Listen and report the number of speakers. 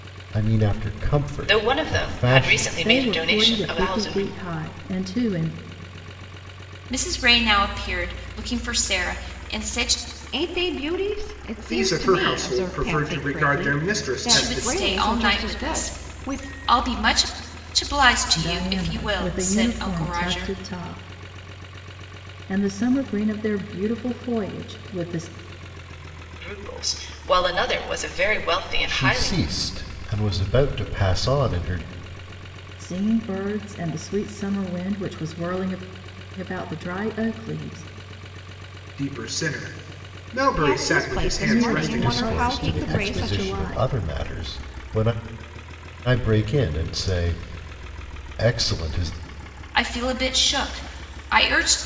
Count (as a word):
six